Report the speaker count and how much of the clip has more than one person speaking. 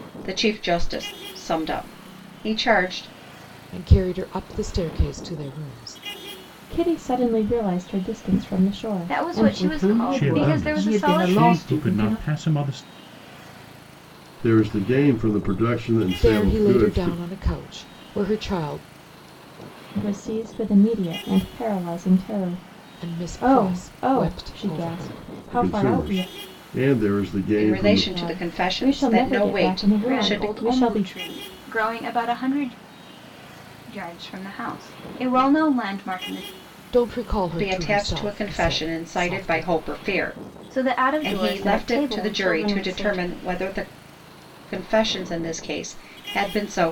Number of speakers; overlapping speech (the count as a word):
seven, about 31%